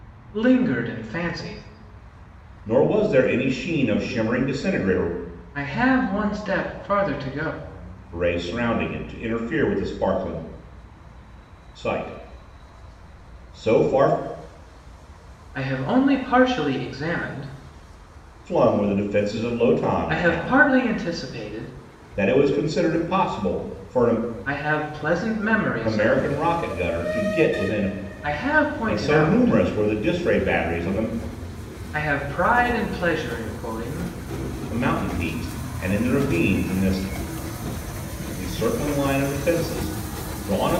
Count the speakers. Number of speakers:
2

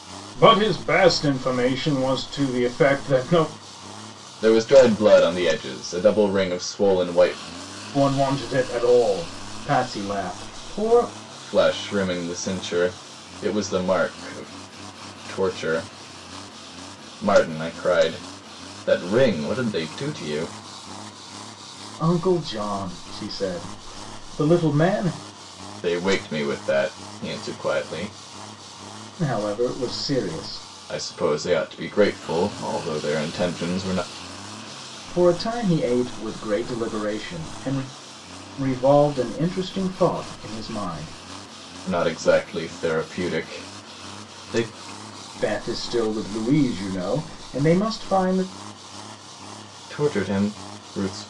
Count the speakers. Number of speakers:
2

